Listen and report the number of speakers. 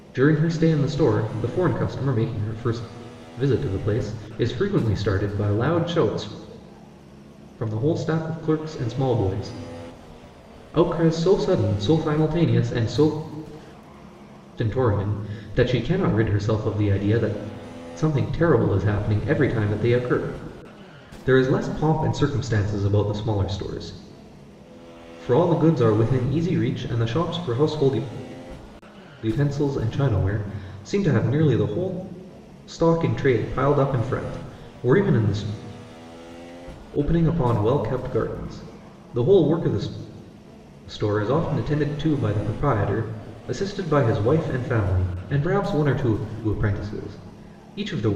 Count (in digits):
1